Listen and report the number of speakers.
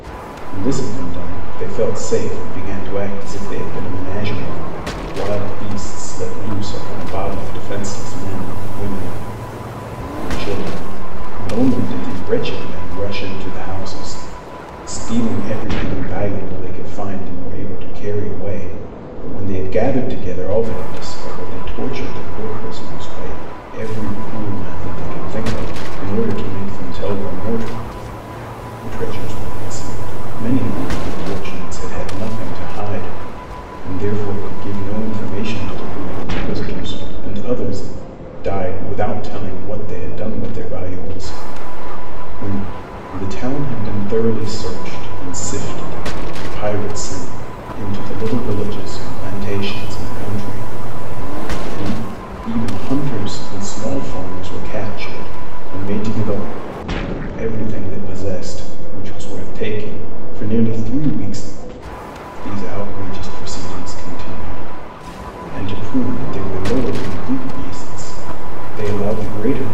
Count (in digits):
1